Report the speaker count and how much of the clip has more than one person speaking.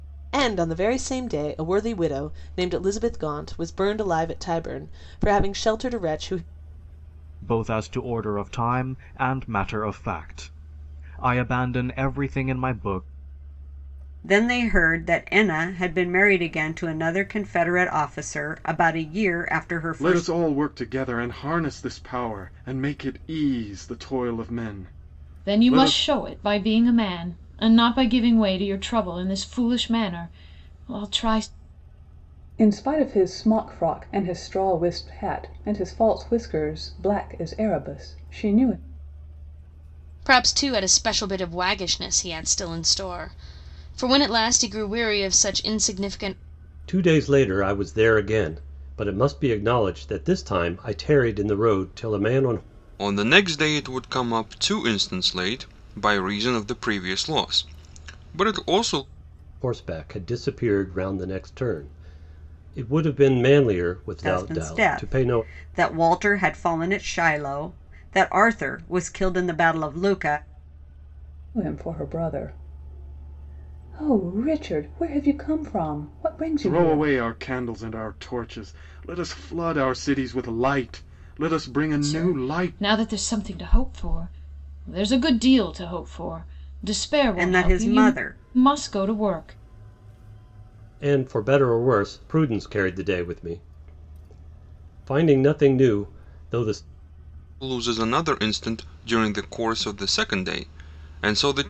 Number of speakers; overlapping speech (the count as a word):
nine, about 4%